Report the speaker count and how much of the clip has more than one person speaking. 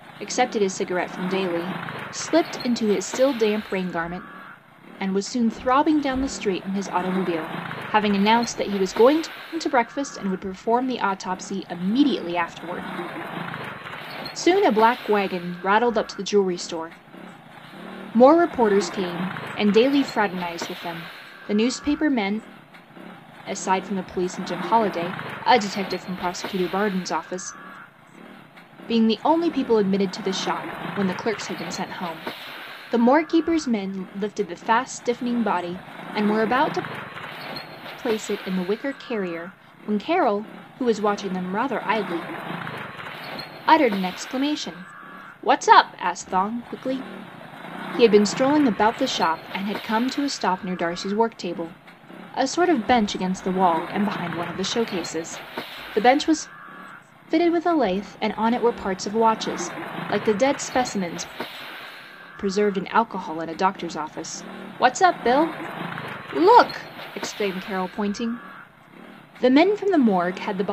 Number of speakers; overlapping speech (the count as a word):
one, no overlap